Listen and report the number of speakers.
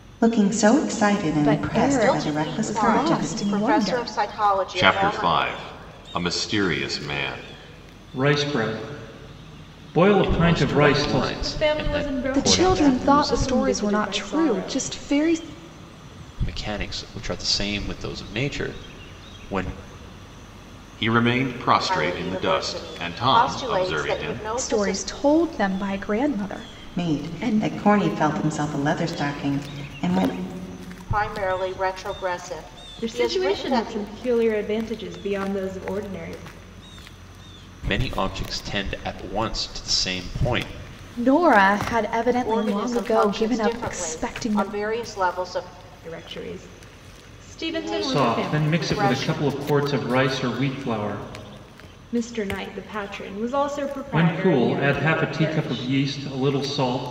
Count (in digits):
7